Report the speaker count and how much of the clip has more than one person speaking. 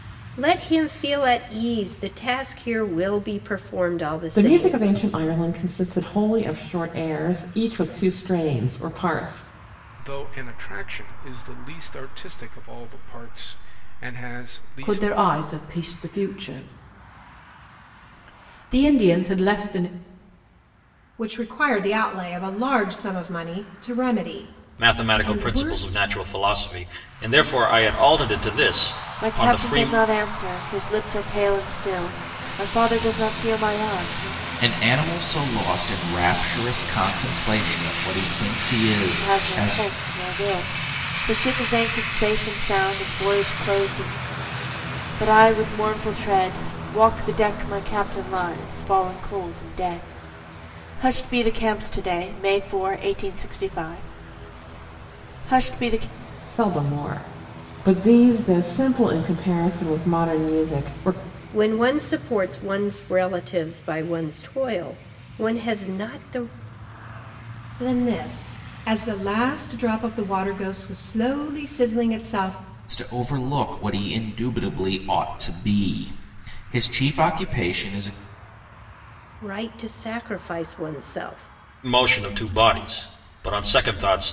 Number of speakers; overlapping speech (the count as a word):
eight, about 4%